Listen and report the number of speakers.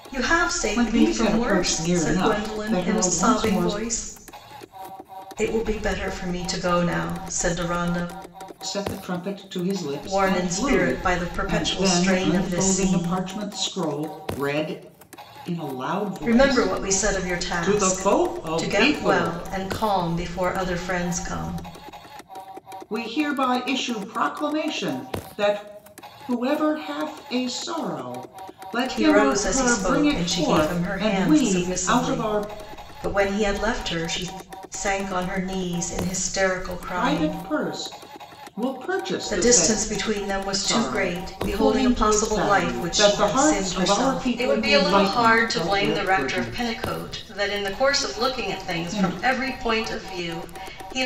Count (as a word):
two